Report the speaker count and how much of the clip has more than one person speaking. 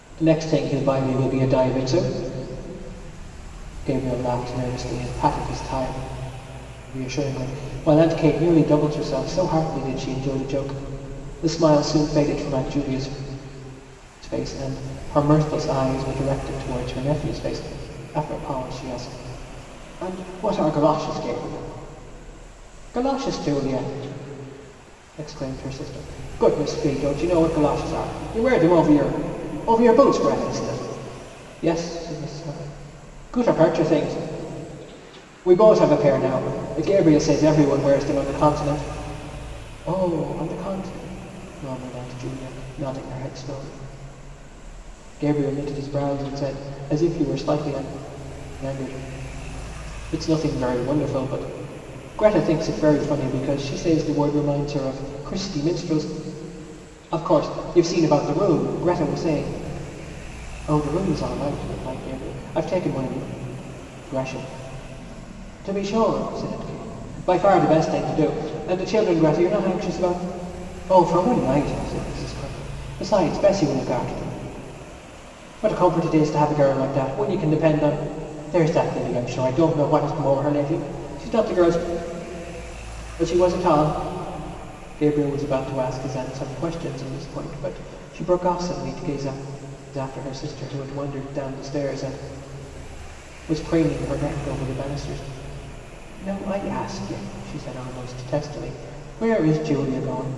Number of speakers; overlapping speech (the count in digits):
1, no overlap